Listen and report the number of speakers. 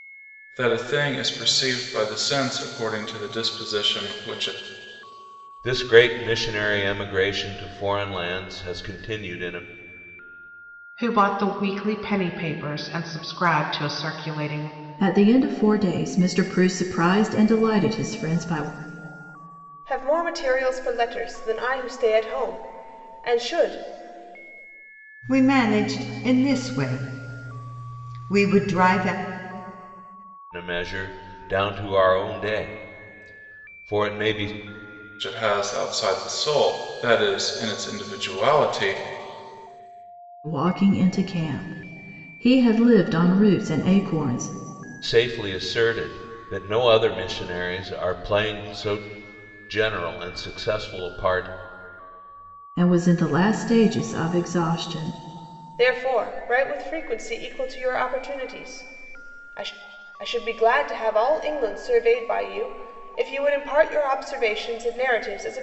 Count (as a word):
six